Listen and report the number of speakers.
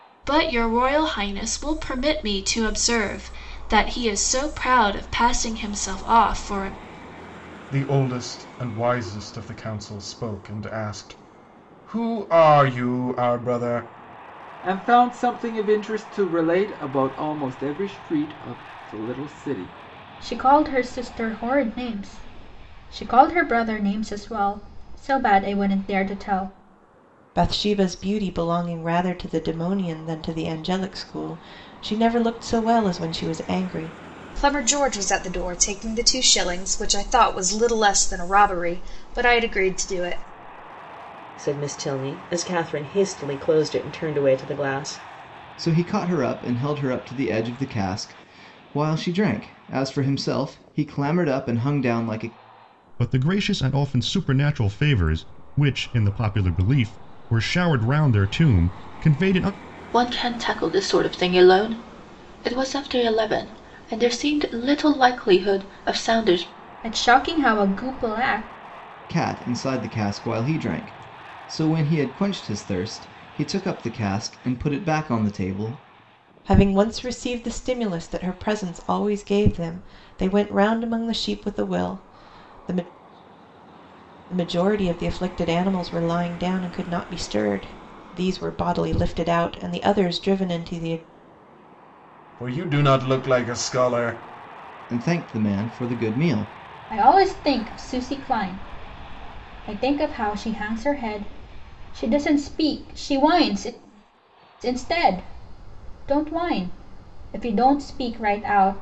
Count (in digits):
10